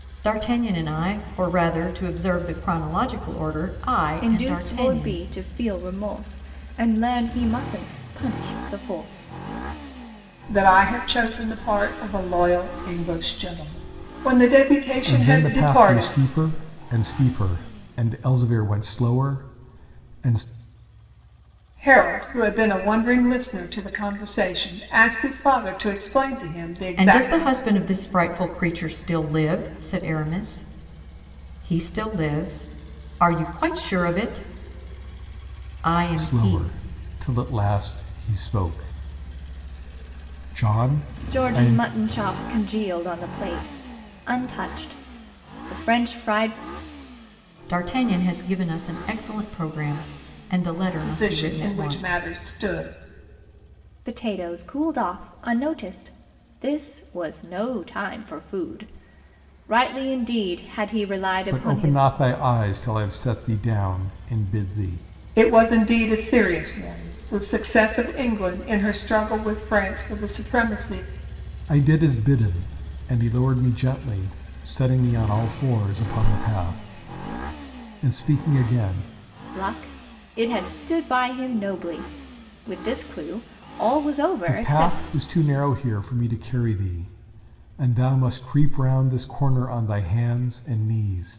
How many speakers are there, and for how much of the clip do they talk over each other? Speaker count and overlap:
4, about 7%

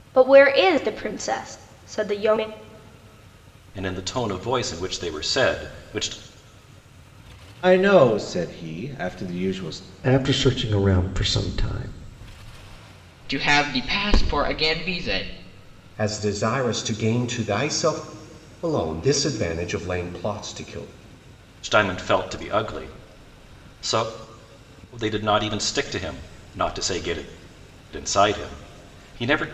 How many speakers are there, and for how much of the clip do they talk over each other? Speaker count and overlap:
6, no overlap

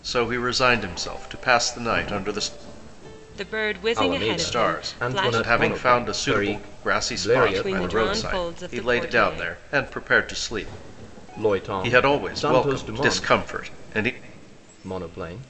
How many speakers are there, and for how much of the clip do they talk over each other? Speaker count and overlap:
3, about 46%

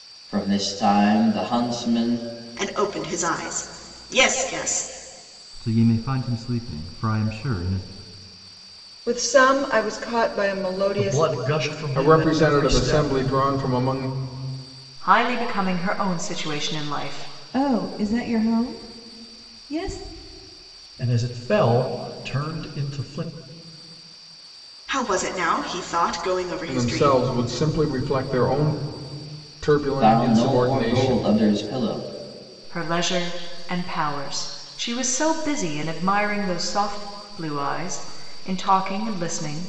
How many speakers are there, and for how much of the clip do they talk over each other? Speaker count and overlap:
8, about 9%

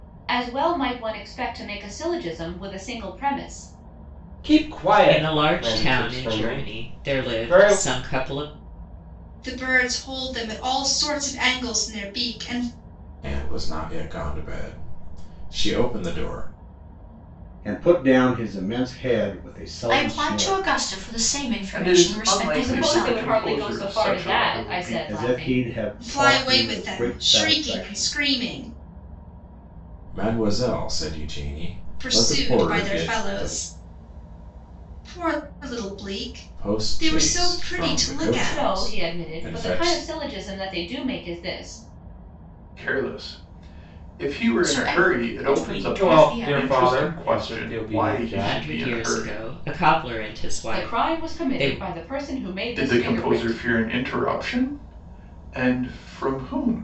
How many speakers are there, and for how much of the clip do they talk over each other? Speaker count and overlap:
8, about 38%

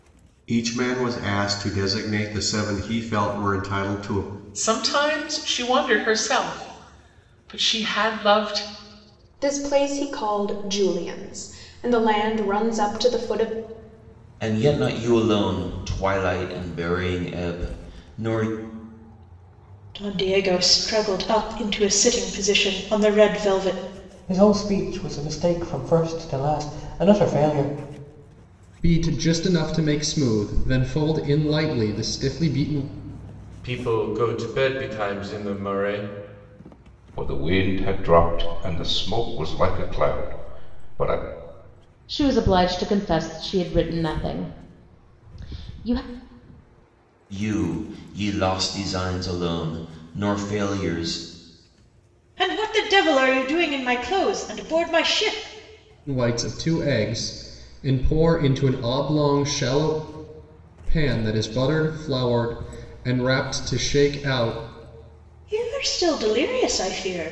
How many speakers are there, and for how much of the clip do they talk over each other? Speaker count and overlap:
10, no overlap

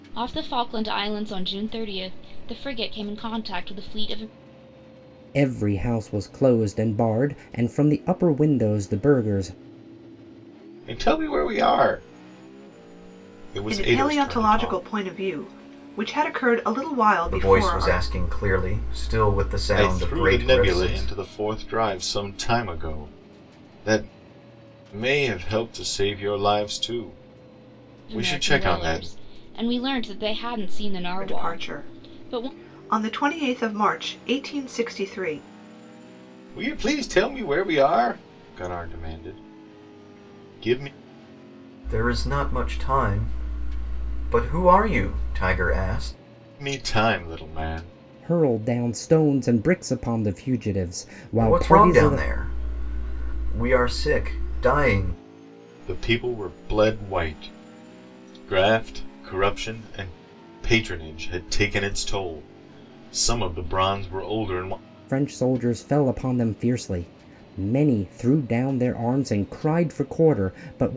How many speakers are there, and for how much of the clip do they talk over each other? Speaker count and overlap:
5, about 9%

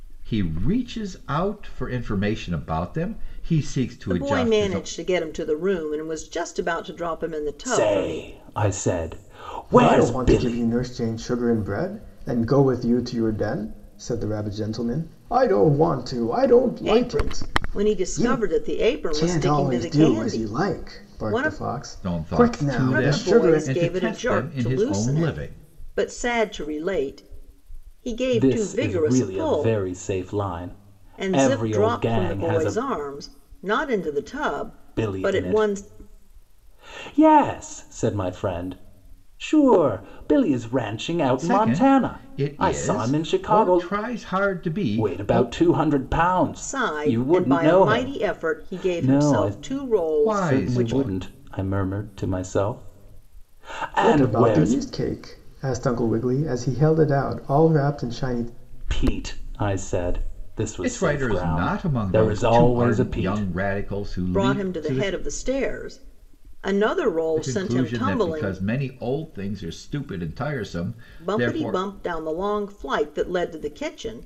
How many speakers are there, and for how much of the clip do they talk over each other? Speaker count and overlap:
4, about 37%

